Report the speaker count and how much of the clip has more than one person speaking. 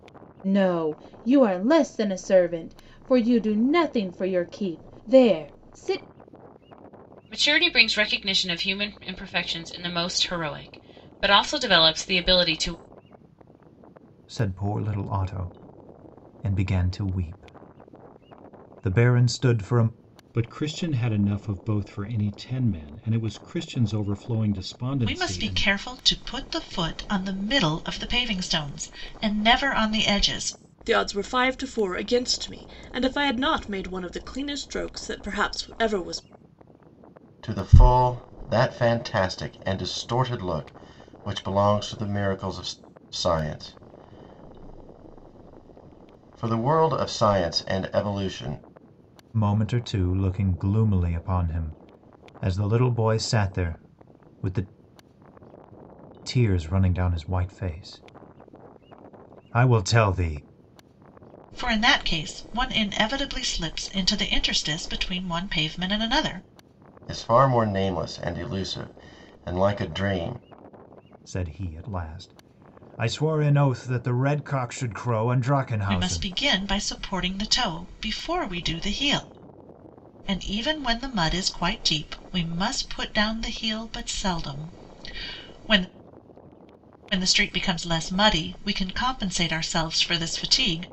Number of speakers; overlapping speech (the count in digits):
7, about 1%